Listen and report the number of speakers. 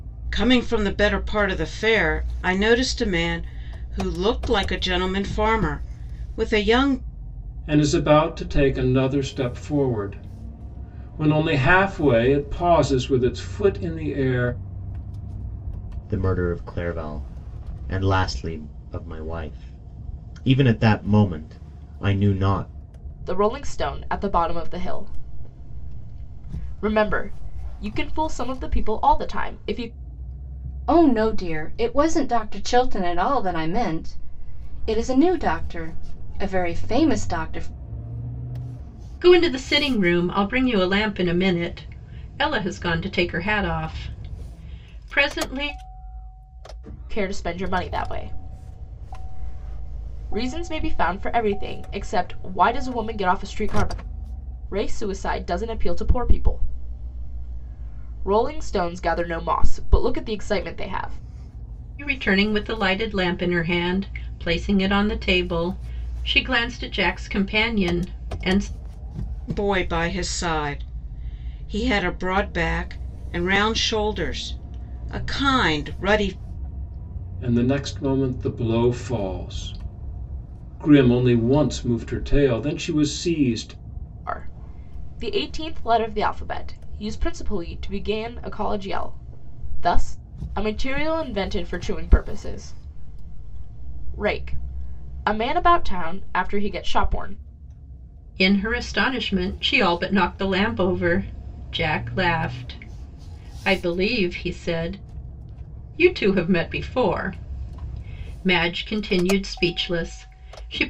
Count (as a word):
six